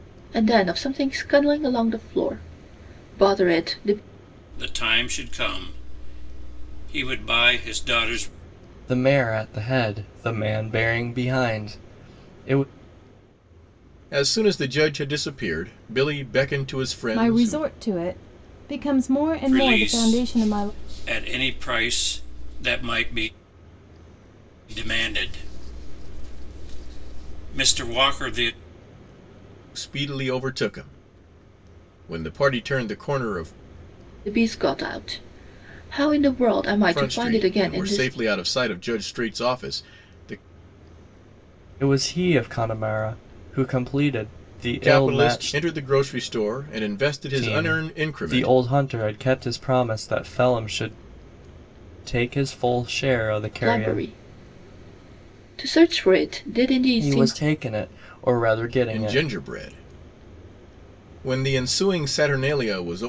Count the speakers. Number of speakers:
5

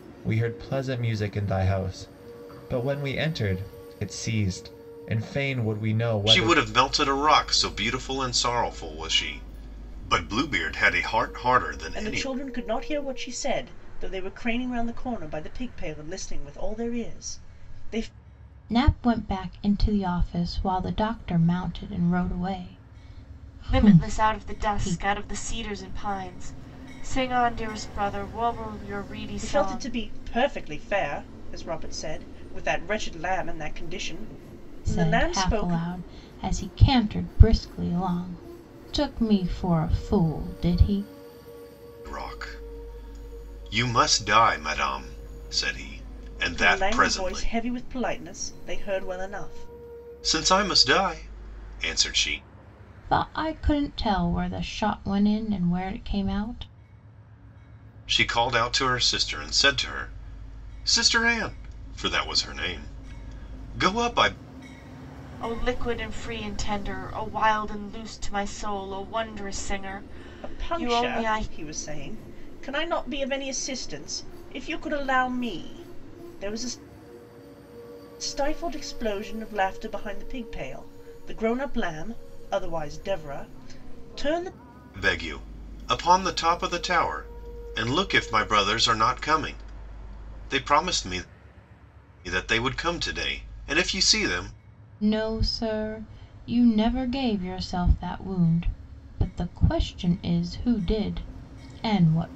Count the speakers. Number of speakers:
5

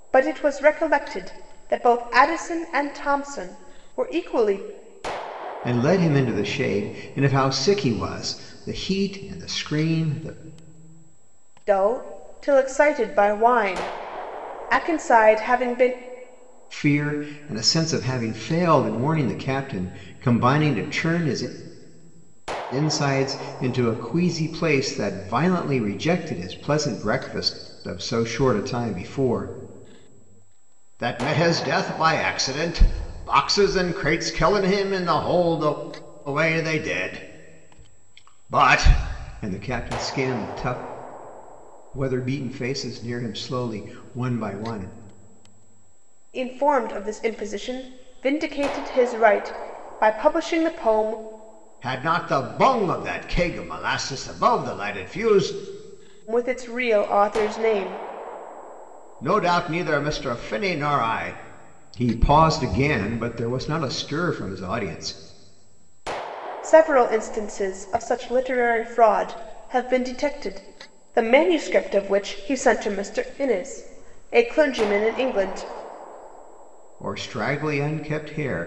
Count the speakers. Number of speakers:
2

